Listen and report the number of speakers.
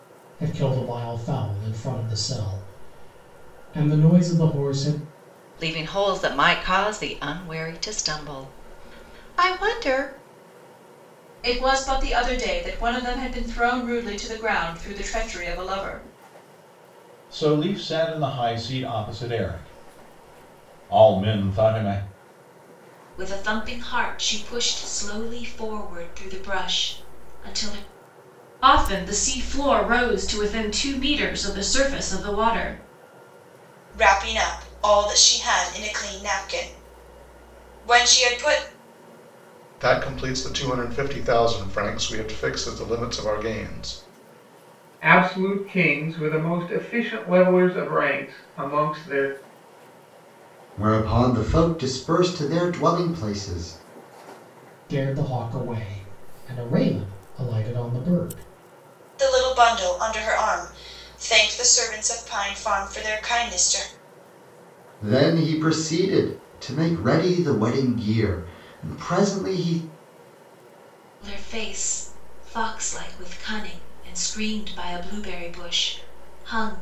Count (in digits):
10